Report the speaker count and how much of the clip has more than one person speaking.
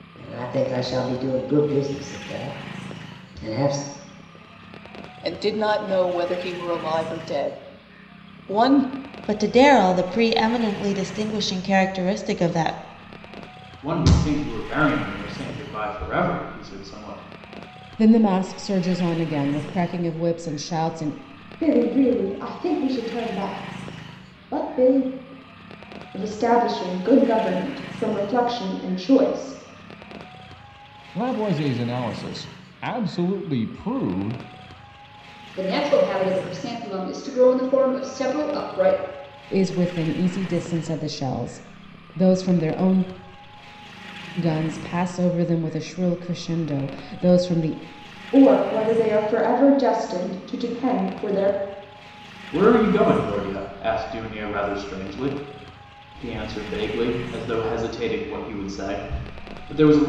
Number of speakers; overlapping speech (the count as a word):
nine, no overlap